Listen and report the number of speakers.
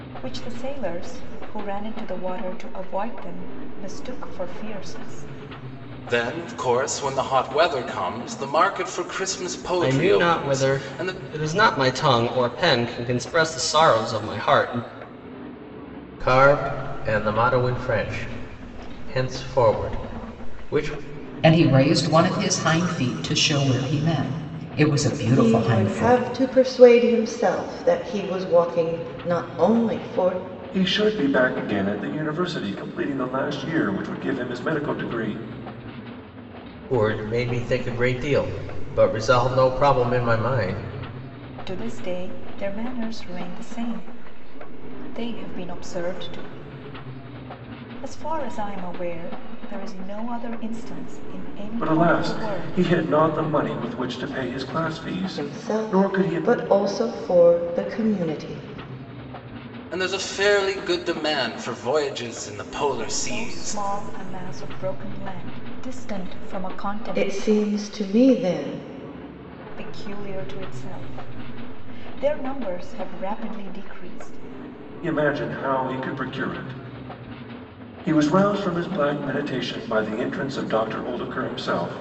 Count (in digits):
7